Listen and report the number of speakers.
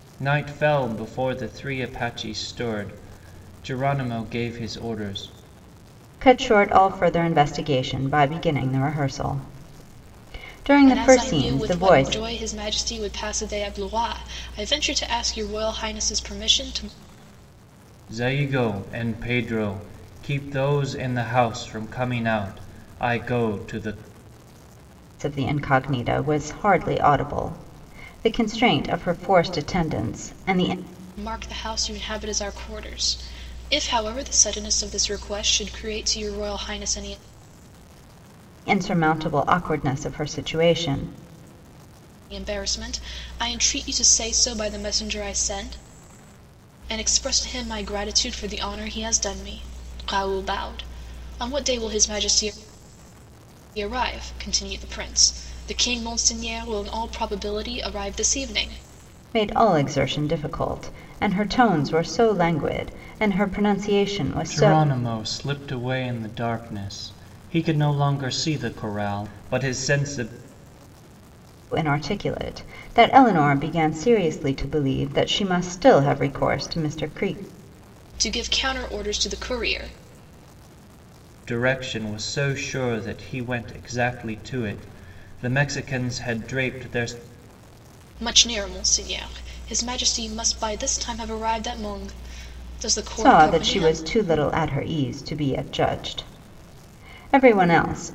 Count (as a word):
three